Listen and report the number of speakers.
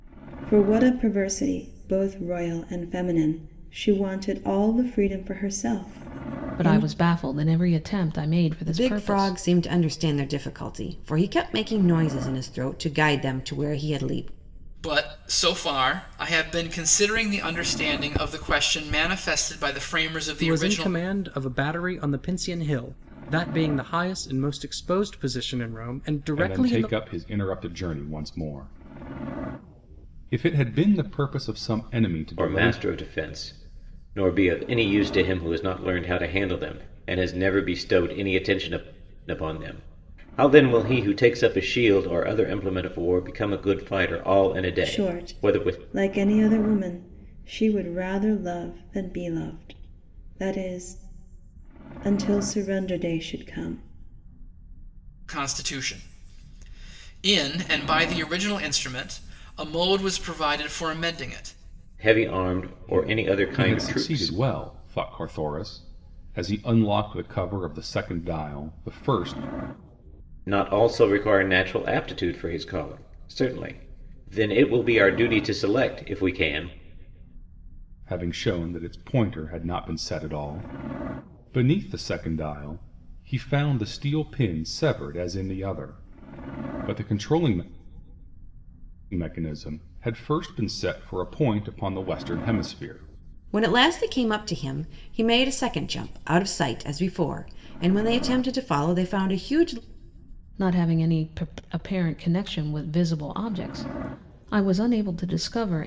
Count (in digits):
7